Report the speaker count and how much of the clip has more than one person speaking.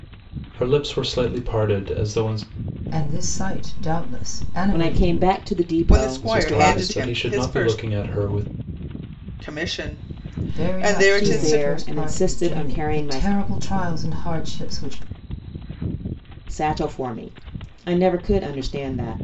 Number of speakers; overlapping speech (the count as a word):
four, about 29%